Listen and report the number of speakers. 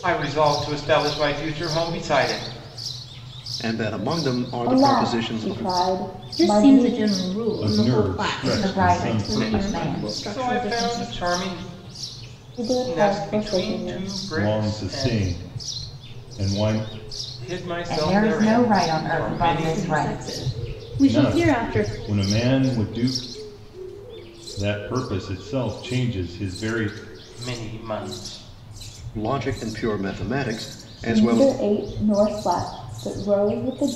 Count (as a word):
six